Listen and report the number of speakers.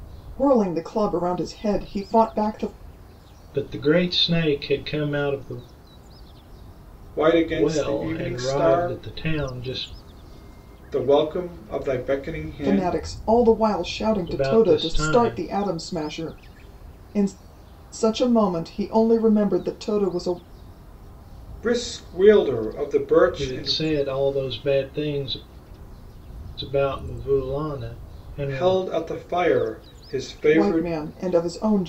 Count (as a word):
three